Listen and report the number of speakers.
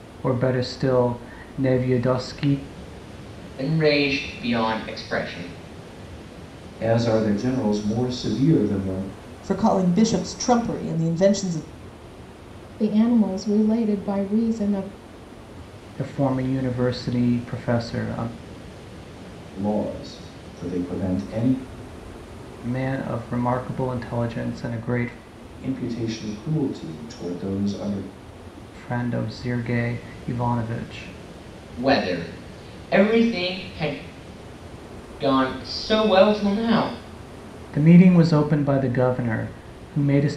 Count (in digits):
5